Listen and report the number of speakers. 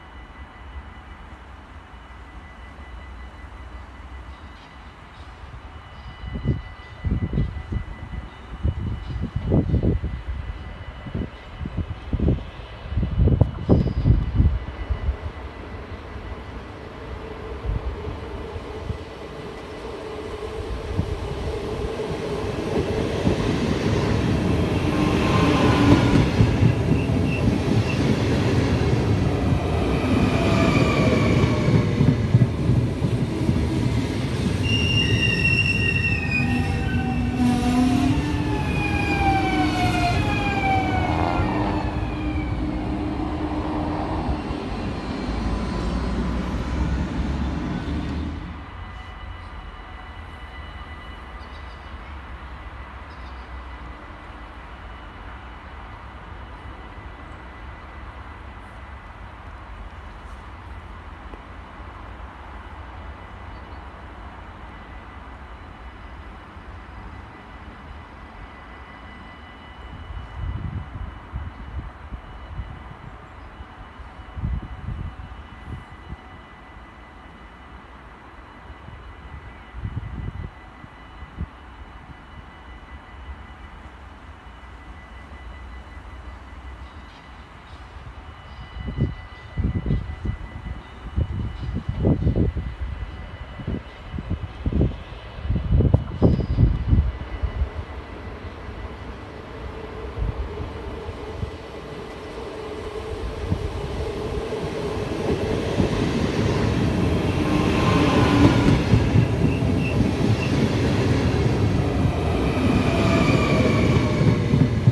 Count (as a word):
zero